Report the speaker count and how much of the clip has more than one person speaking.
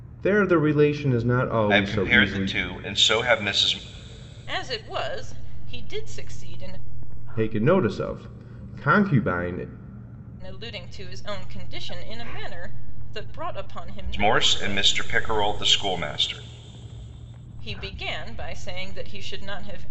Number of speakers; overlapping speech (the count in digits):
3, about 9%